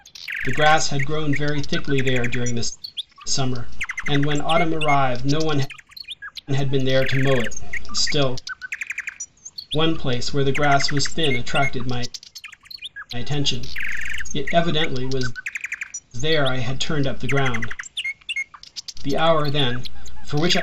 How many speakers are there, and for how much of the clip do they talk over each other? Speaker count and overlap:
one, no overlap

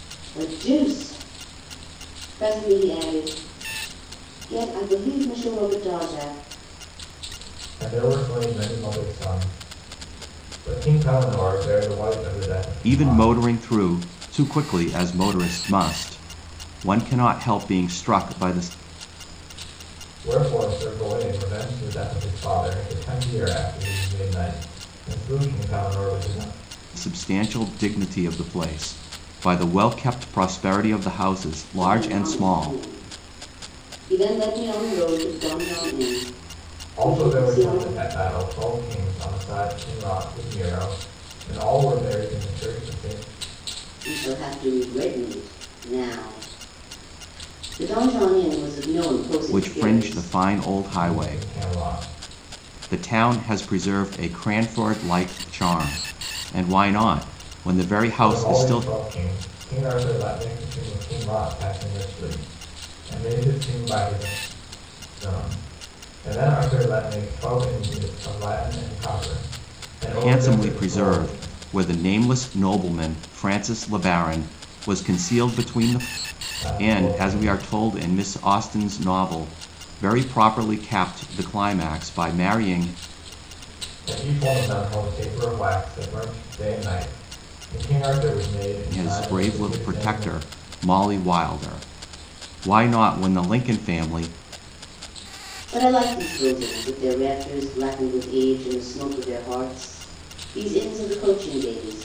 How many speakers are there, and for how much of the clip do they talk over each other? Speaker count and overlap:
three, about 8%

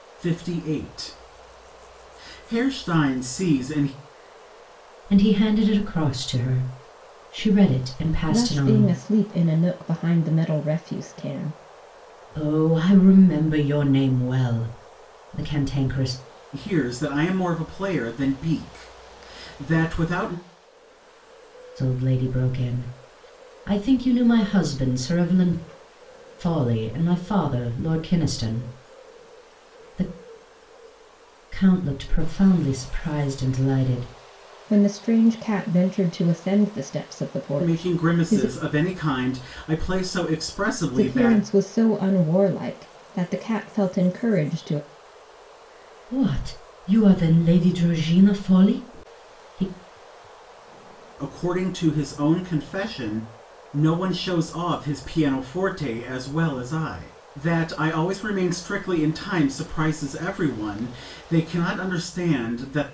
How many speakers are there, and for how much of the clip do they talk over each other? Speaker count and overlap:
three, about 3%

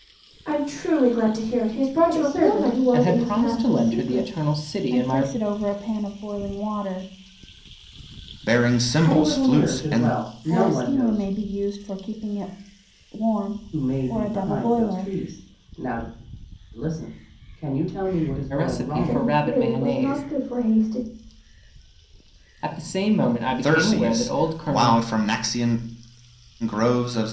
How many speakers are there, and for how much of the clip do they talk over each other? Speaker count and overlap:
six, about 35%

